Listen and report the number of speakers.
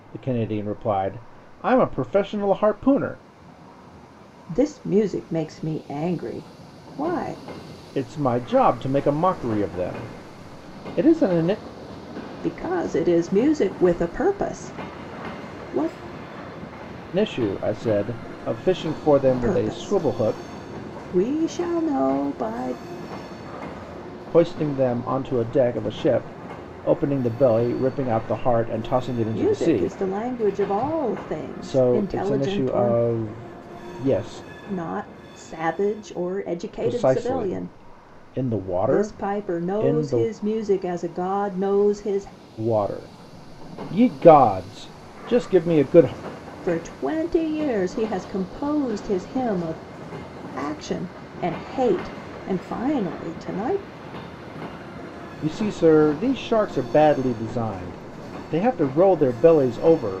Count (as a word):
two